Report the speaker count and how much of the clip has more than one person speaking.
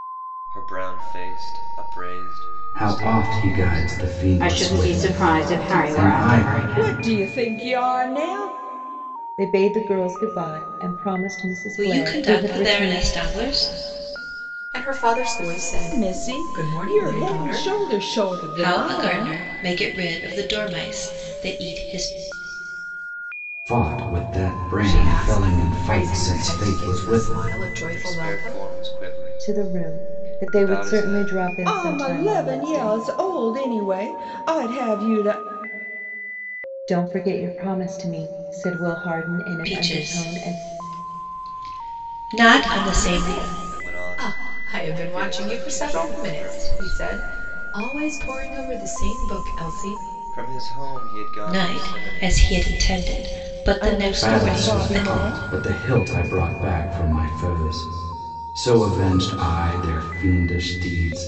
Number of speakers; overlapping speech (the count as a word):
seven, about 37%